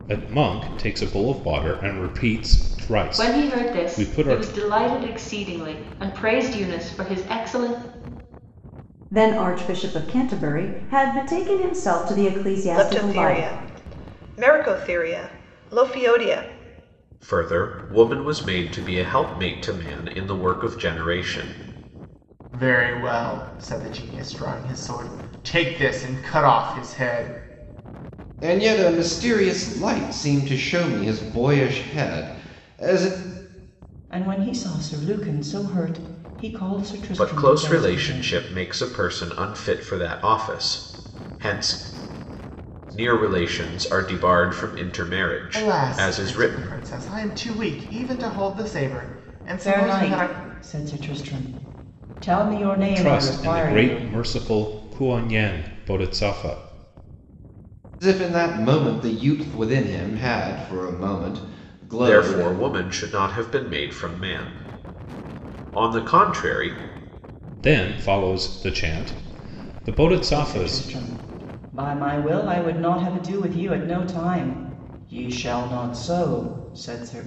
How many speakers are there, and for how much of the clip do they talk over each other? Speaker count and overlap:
8, about 10%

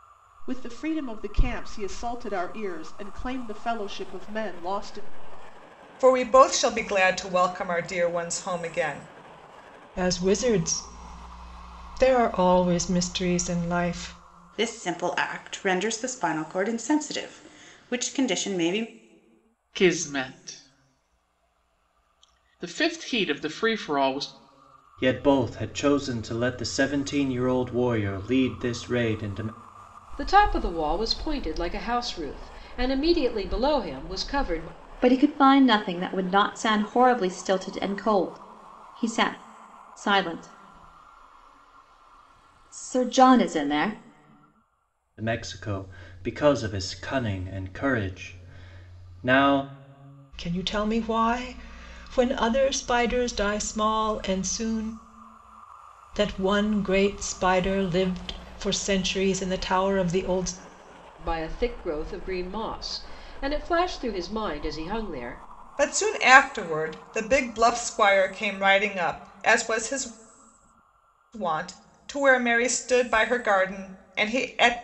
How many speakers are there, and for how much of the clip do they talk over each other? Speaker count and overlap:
8, no overlap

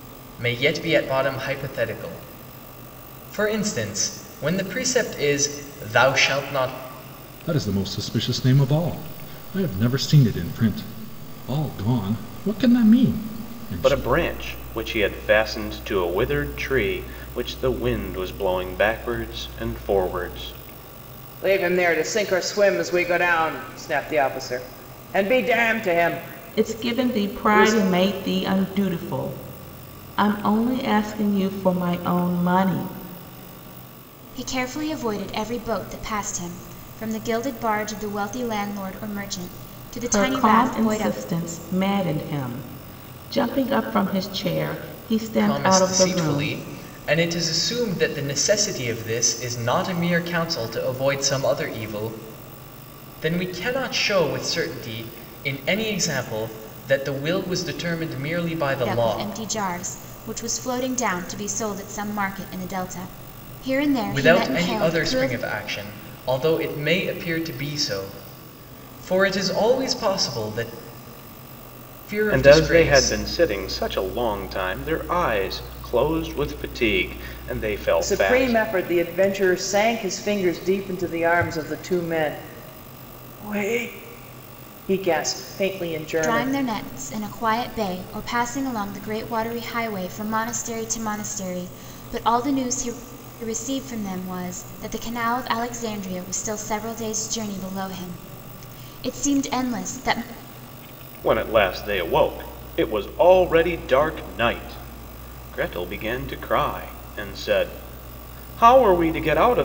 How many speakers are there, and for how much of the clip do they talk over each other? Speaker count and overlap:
6, about 7%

